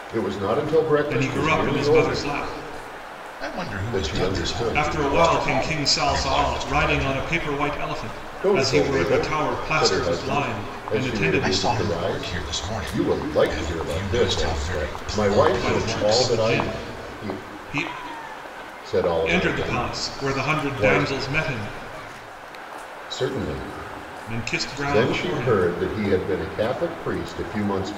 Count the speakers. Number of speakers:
3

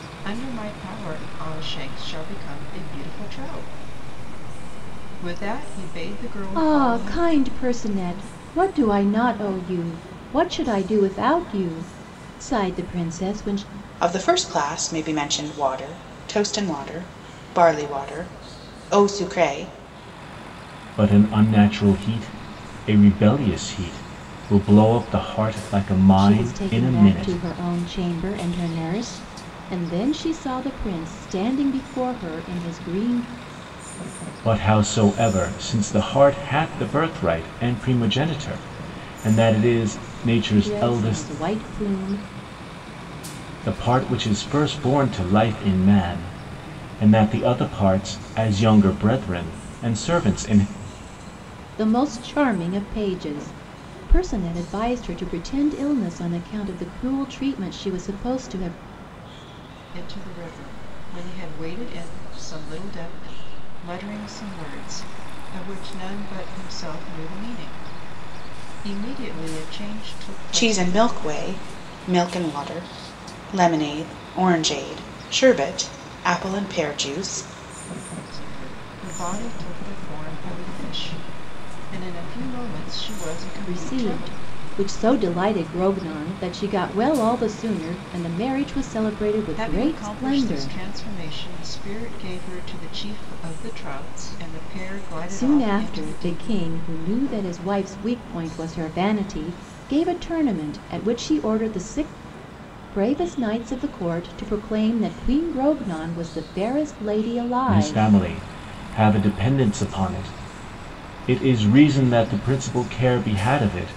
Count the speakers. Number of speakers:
4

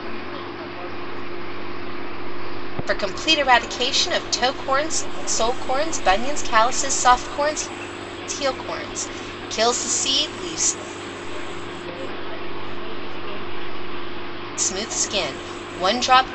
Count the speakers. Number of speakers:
2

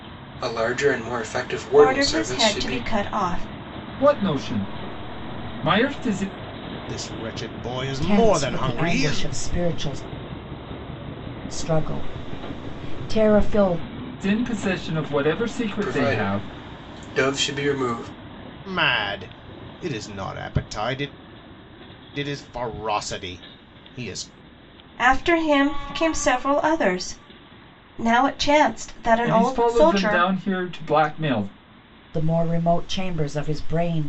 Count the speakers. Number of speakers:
5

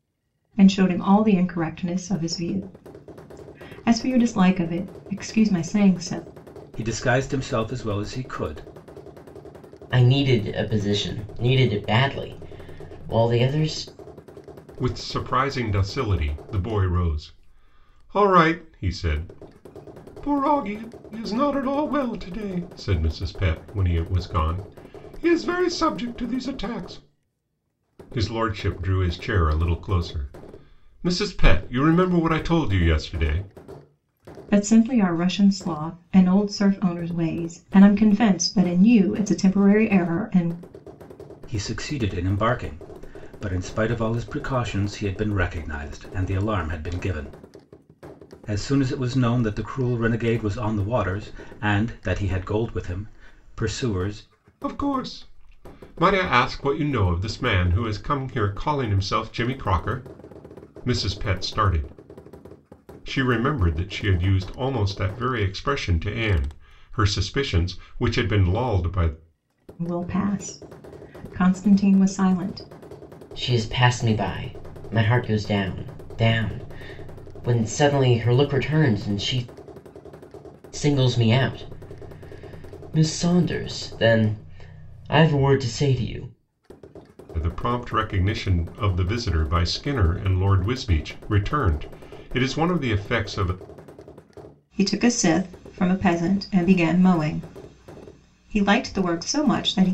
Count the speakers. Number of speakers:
4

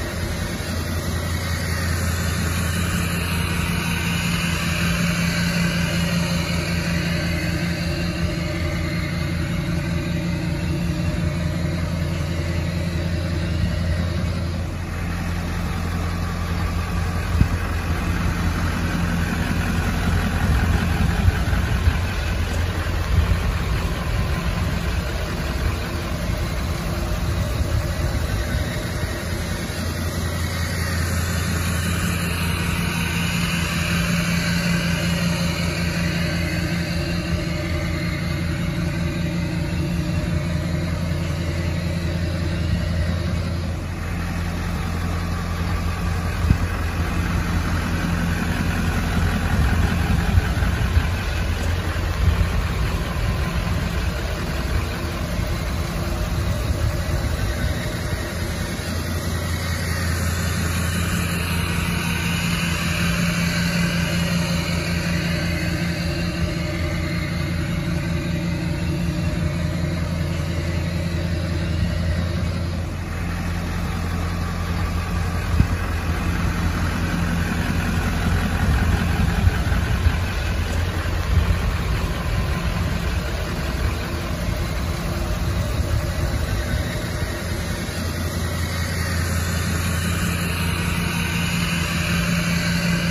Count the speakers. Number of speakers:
0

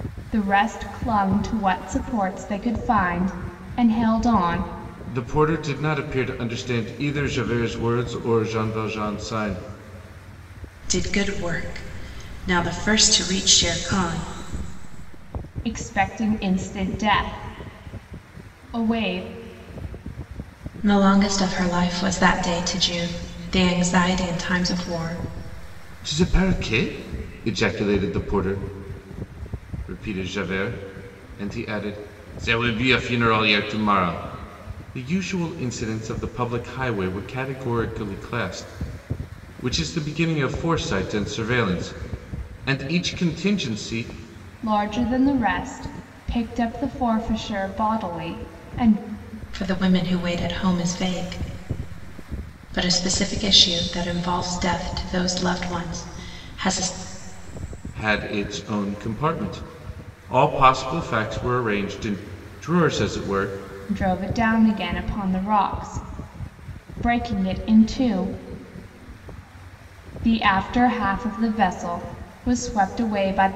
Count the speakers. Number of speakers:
3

